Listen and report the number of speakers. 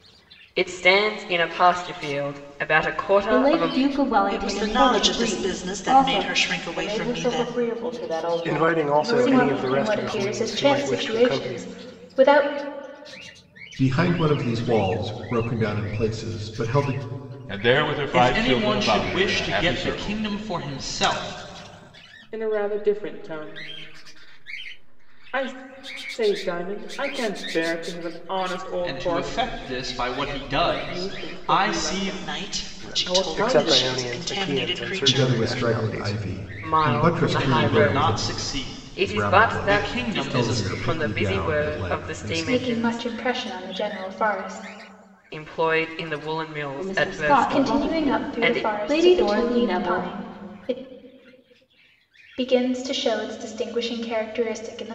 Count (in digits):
10